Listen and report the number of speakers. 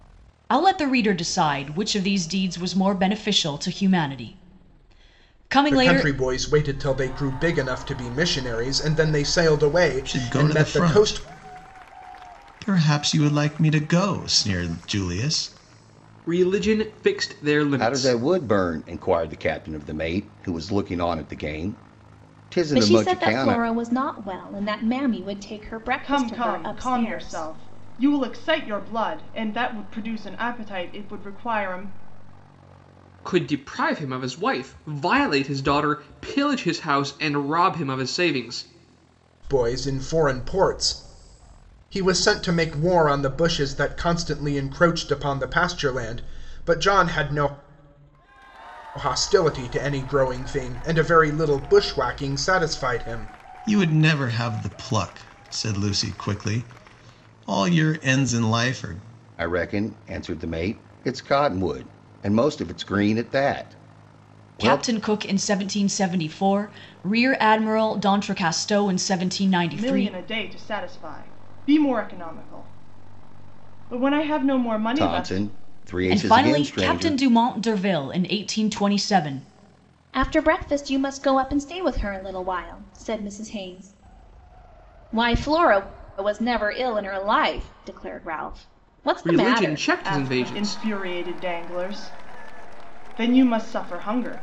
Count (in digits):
7